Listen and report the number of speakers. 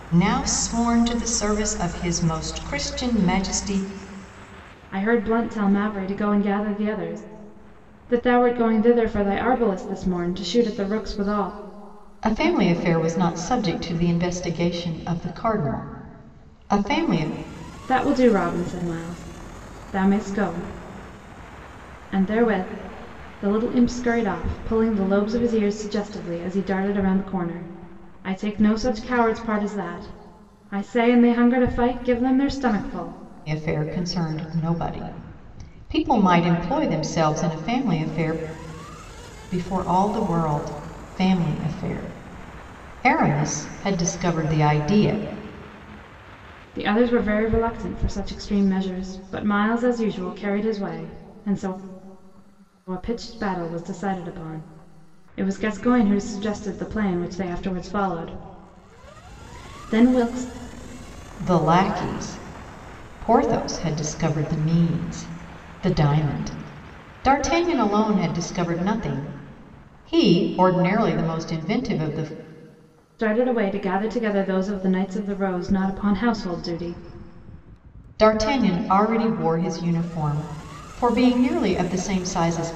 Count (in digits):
2